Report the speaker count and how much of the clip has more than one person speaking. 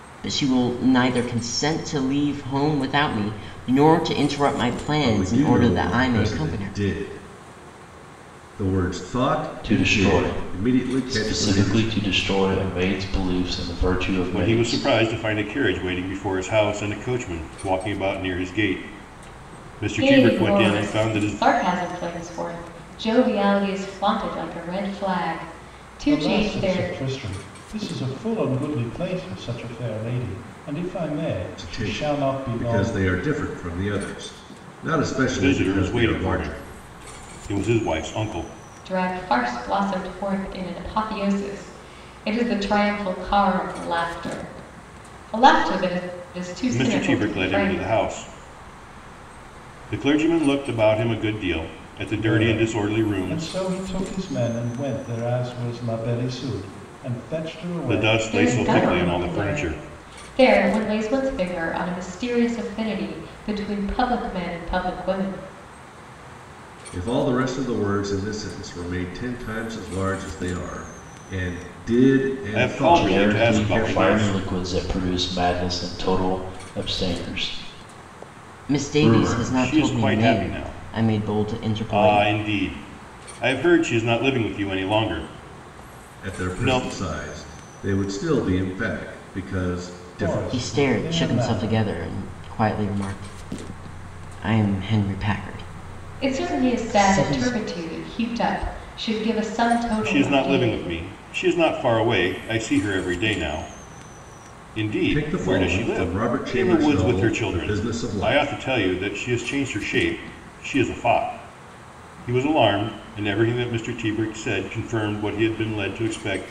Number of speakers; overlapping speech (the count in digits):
6, about 24%